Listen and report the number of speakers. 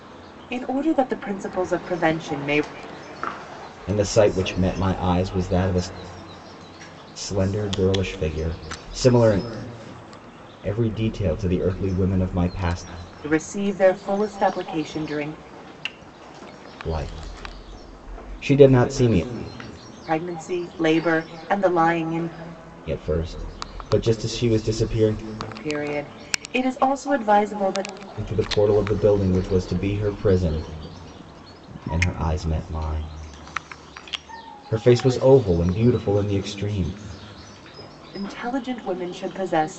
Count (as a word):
two